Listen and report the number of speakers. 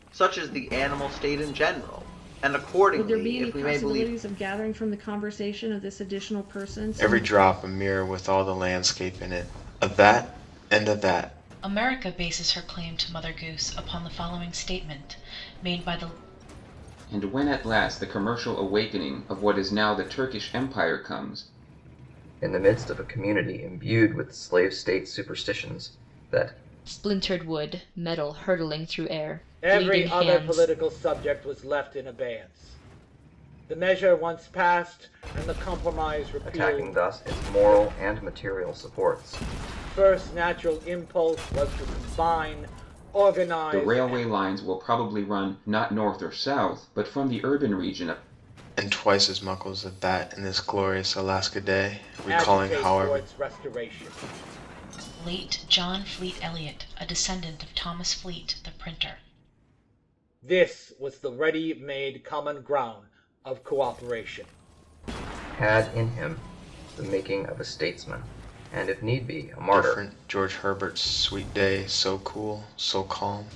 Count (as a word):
eight